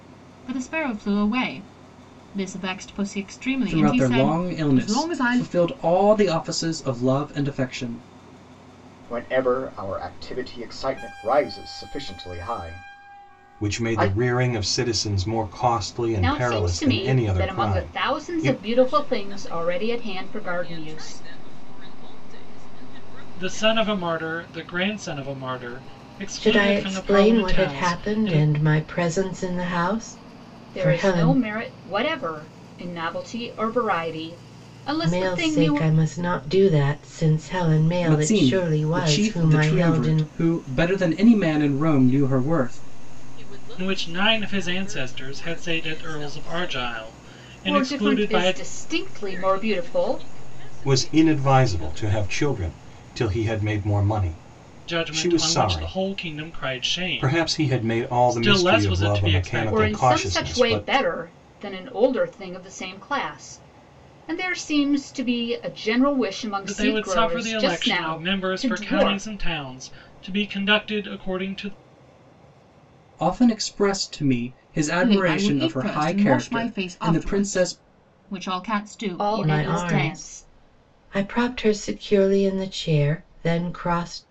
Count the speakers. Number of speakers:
eight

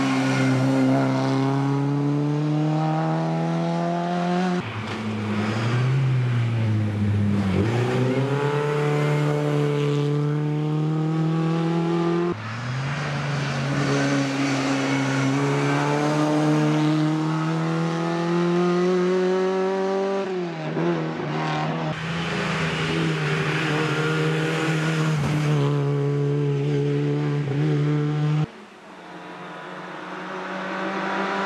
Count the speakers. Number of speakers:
zero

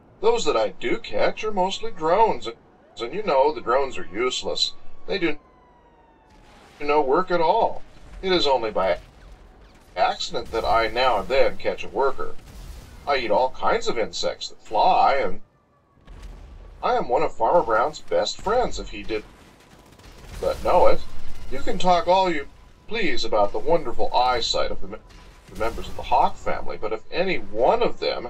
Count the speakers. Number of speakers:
one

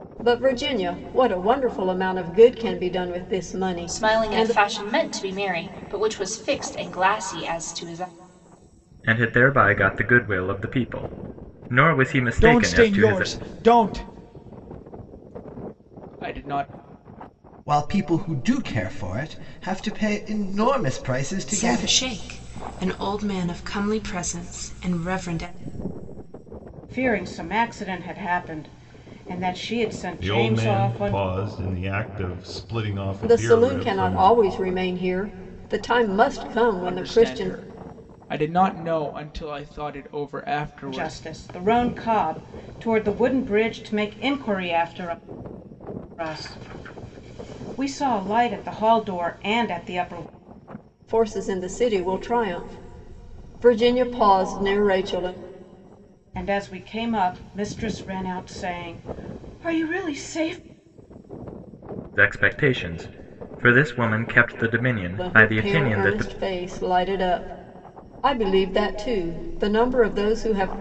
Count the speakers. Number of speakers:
eight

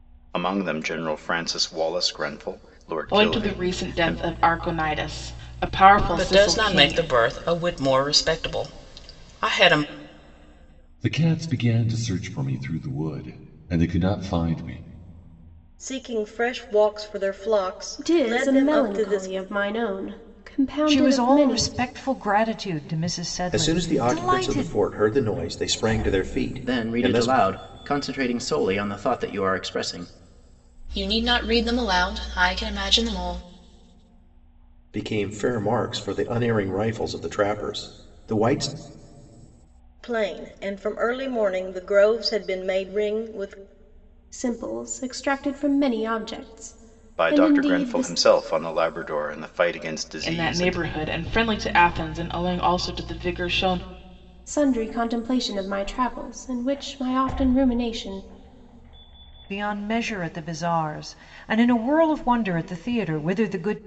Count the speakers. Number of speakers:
ten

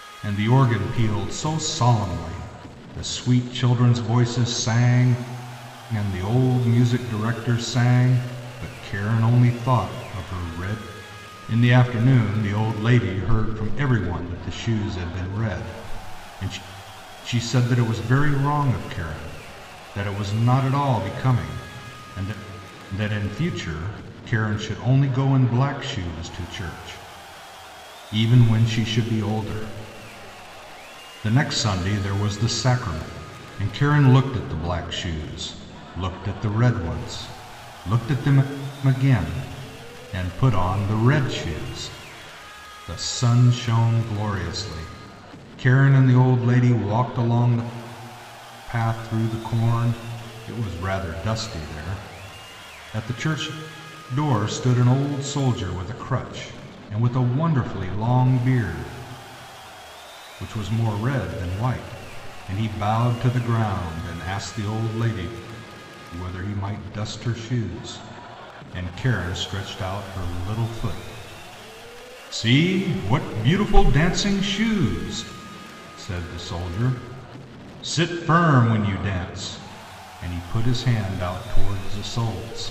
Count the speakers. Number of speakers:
one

